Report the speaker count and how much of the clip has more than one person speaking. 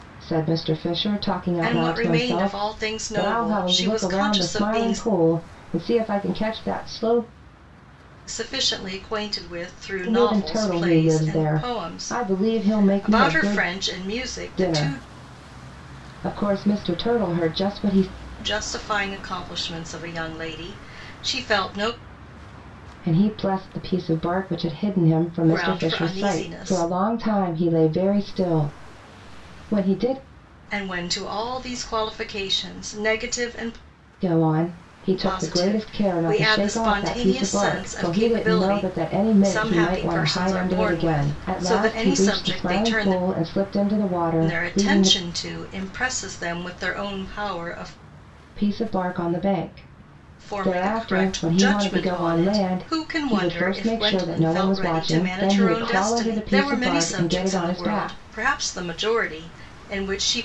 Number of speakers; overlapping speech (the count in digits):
2, about 41%